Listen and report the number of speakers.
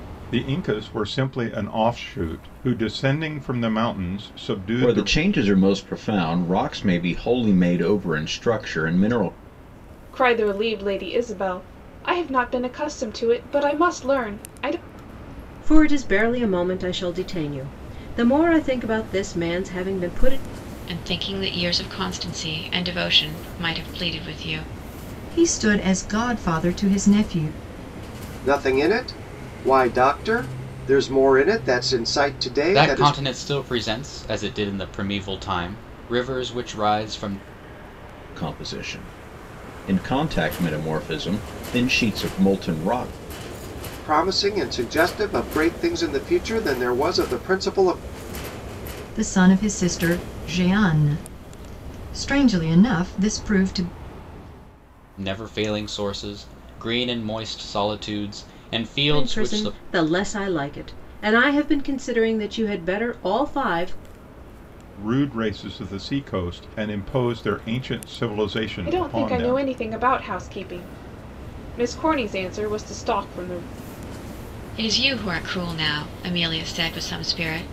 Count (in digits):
8